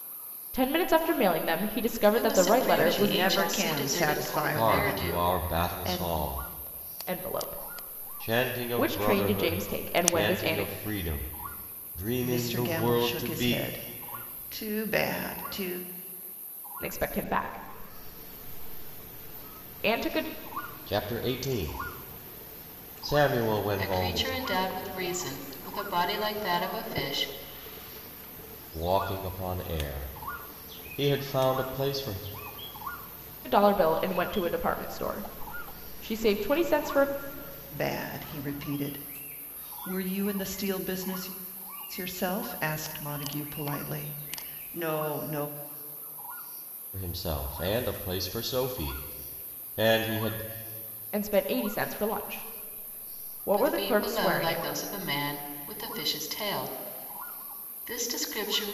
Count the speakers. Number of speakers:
four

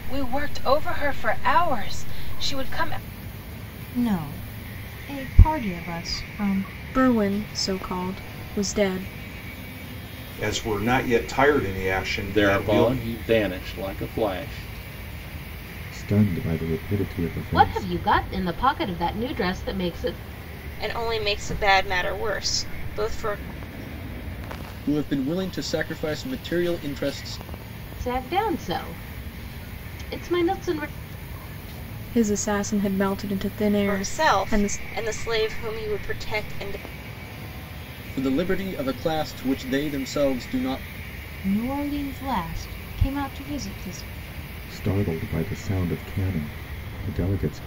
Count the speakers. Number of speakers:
nine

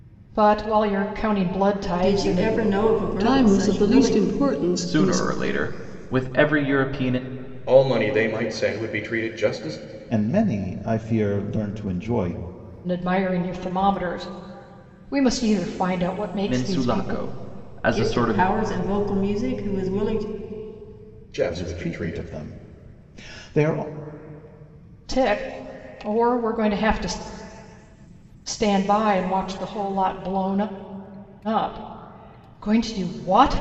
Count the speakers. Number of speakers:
six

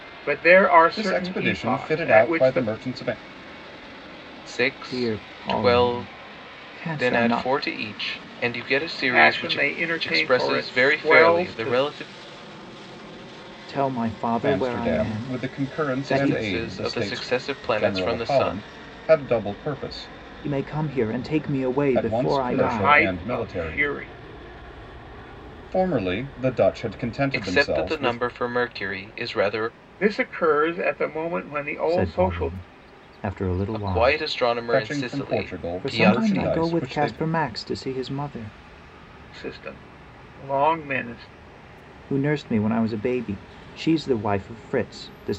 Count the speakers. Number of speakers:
four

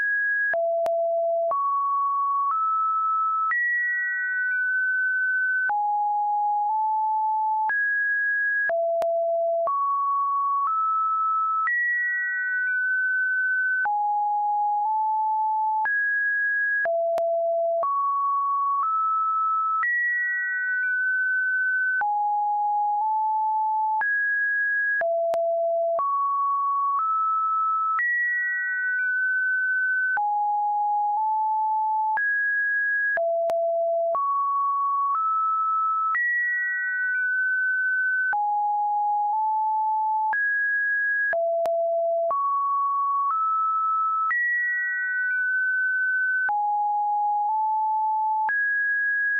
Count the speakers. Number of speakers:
zero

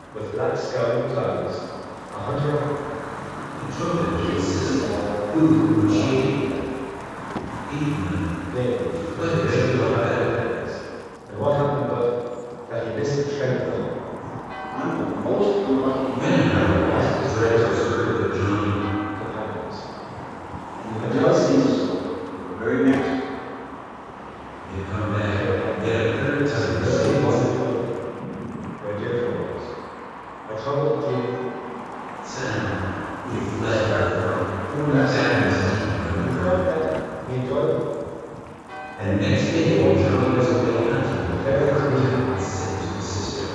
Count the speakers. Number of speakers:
three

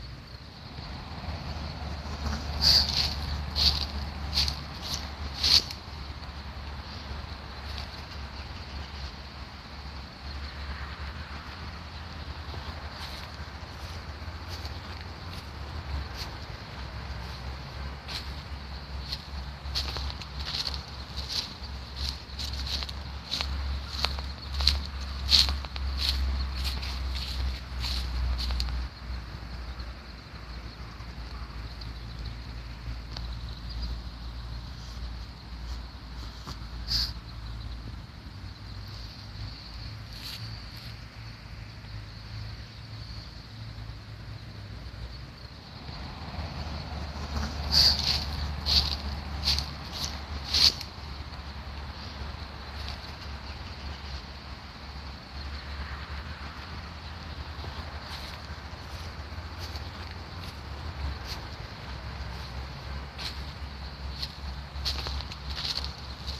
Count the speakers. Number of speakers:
zero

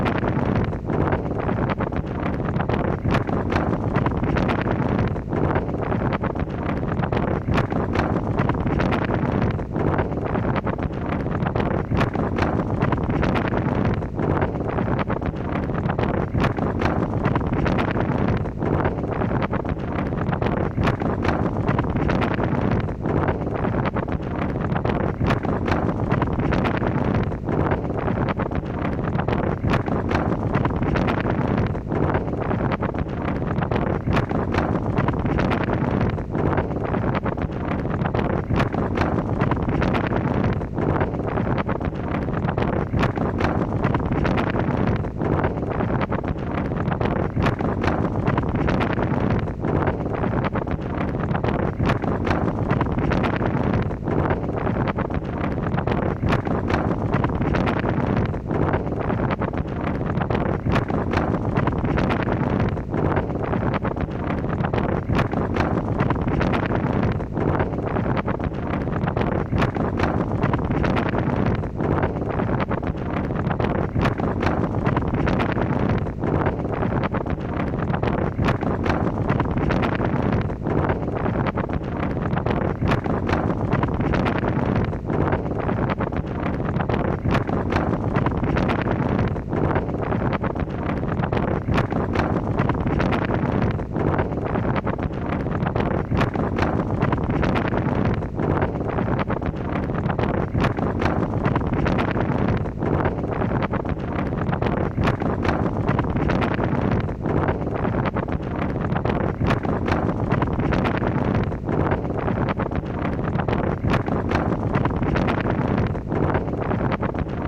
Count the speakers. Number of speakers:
zero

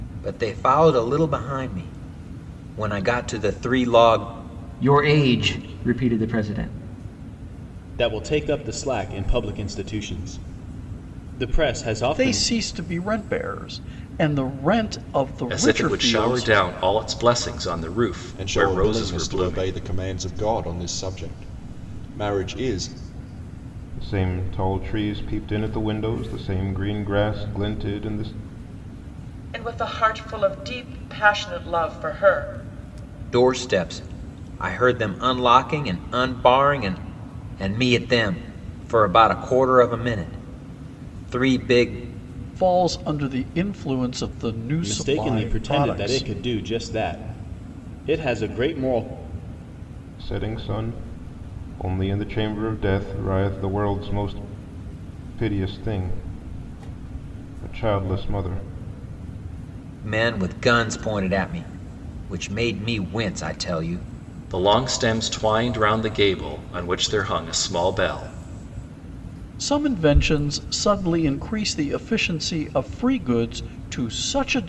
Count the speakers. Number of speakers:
eight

